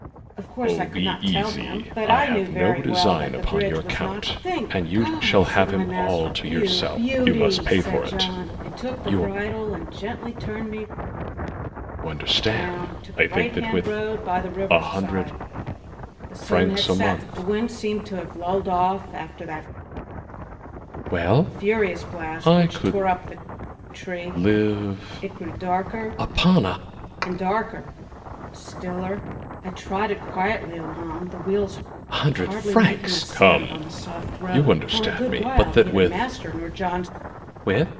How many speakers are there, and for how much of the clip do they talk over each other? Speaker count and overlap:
two, about 54%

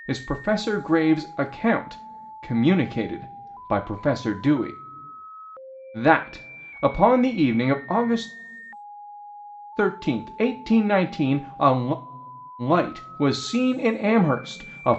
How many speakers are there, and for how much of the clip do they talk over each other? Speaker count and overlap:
one, no overlap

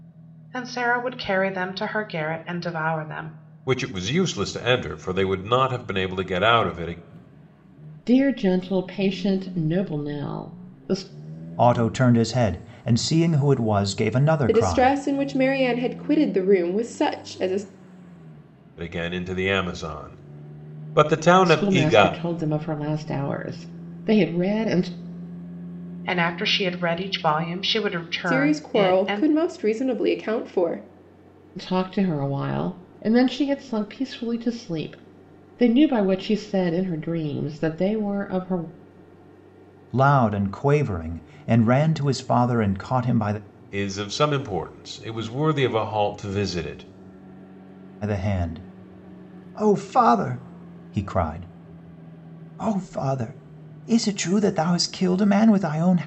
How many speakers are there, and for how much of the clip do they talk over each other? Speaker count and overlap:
five, about 4%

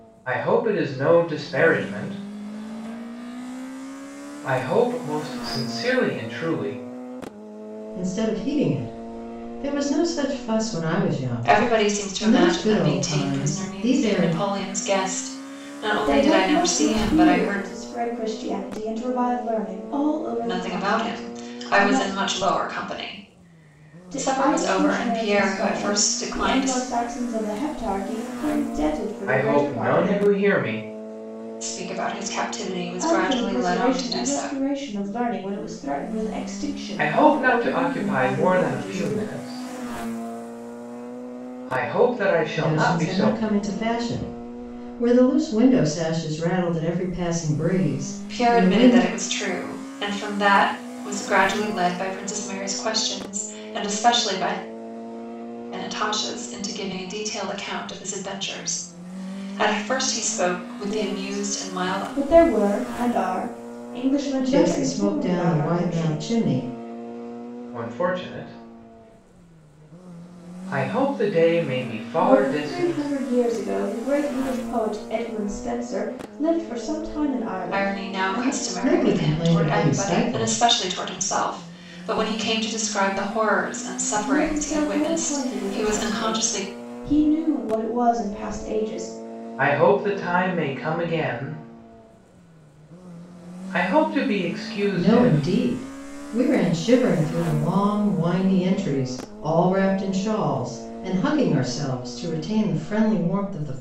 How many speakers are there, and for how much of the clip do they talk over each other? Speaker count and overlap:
four, about 24%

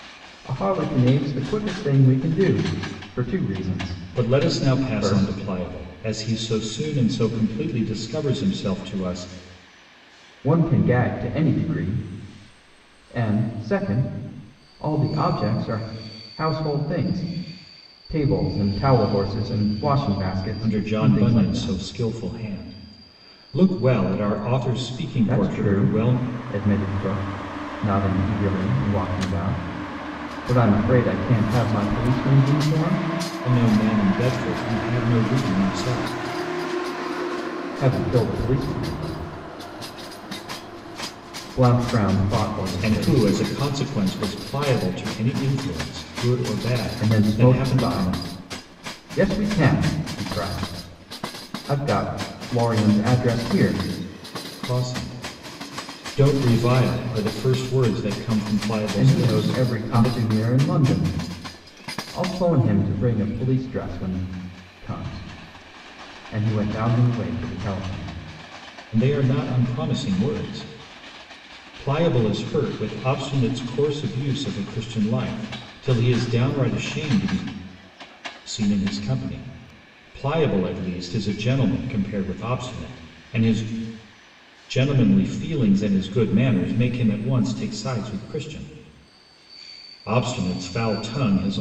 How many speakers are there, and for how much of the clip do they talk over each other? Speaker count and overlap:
two, about 7%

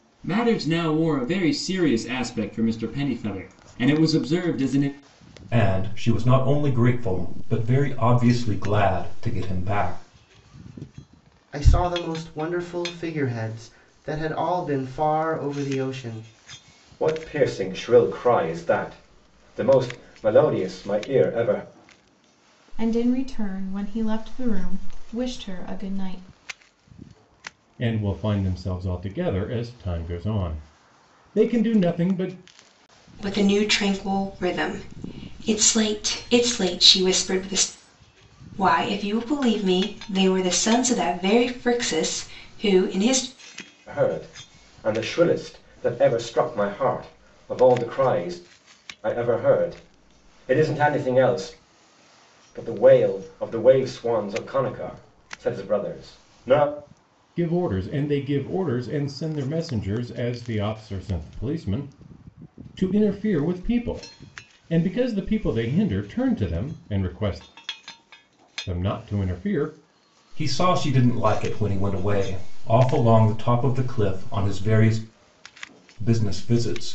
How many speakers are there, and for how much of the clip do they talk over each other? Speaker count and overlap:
seven, no overlap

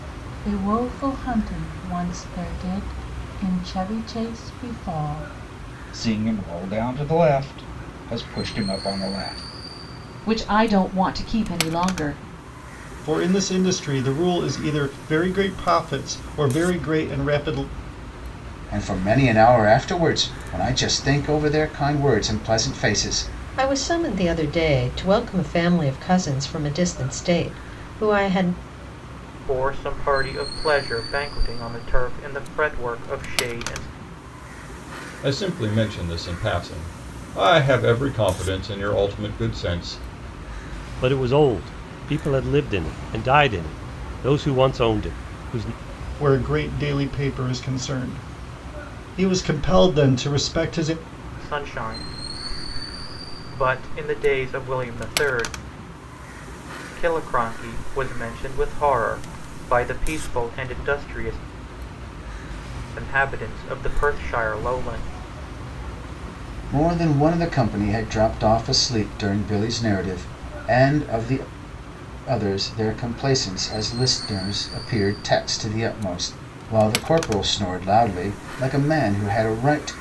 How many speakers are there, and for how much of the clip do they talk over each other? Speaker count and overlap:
nine, no overlap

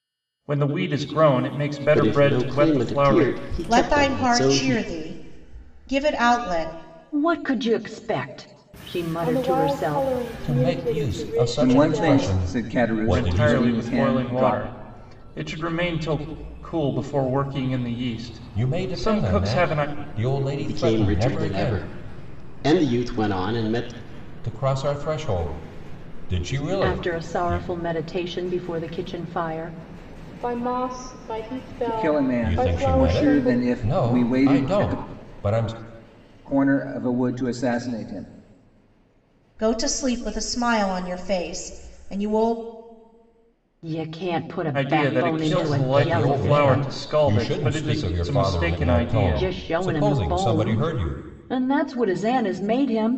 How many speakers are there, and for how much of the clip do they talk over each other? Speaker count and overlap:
seven, about 40%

